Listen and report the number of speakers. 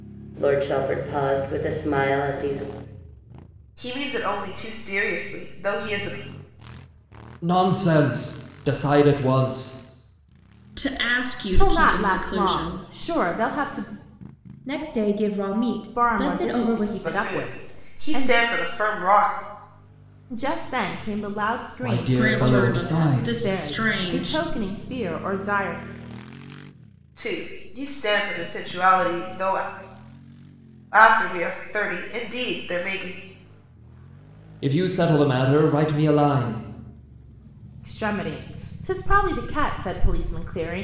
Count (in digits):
6